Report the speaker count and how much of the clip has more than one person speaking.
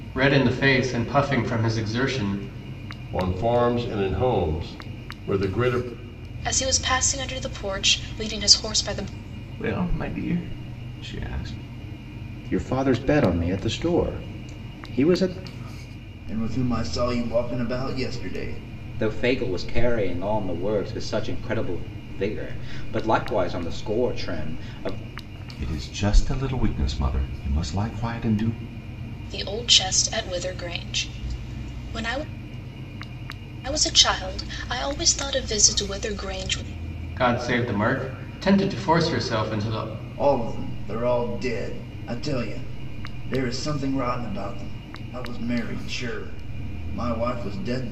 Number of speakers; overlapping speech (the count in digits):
7, no overlap